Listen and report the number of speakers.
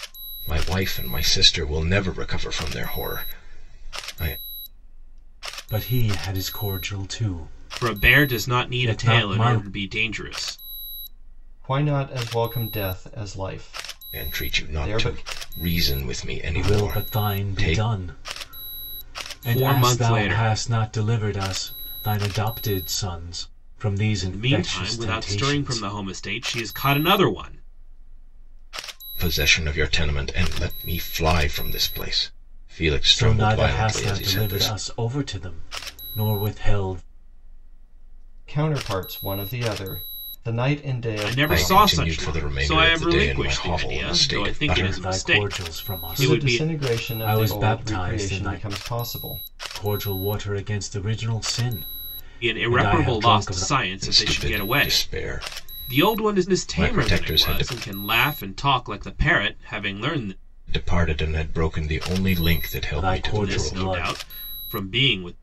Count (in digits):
4